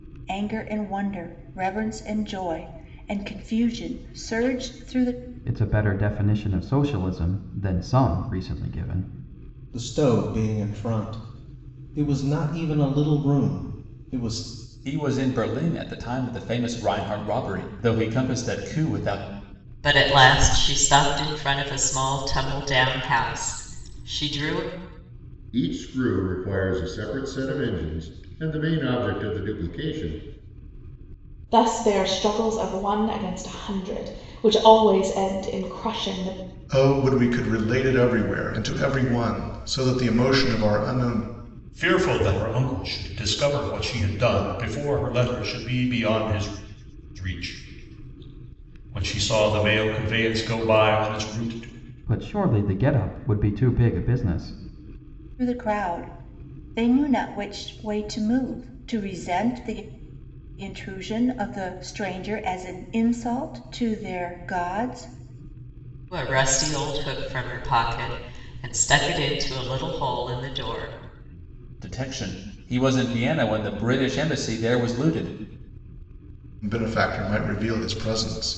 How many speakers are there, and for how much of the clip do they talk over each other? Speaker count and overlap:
9, no overlap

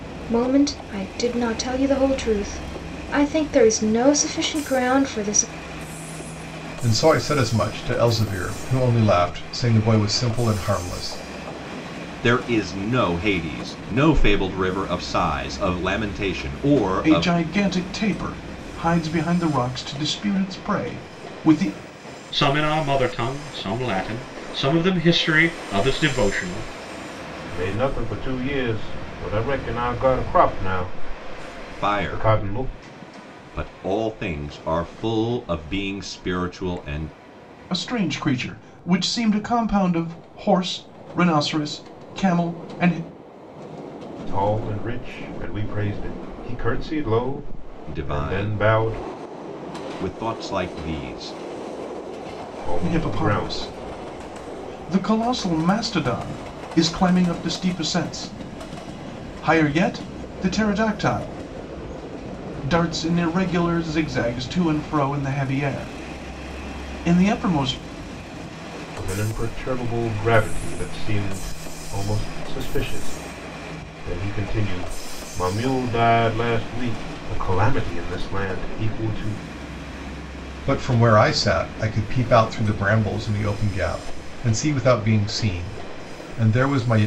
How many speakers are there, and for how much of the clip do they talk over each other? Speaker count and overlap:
6, about 4%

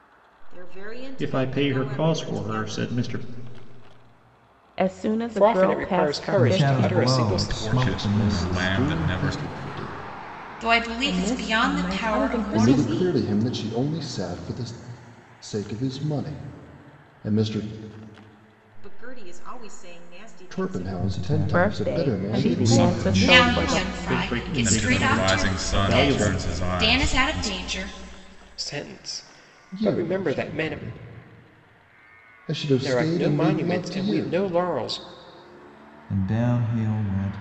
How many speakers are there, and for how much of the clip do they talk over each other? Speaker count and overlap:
9, about 48%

